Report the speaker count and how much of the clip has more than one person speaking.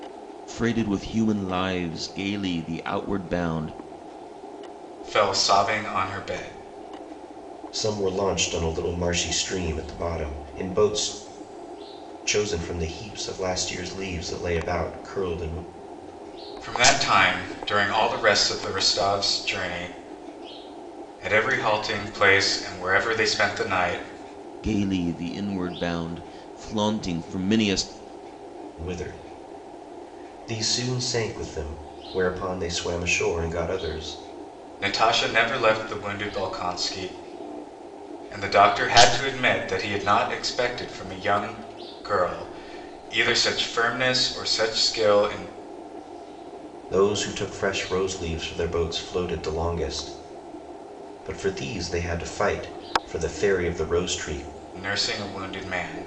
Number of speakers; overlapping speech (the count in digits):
3, no overlap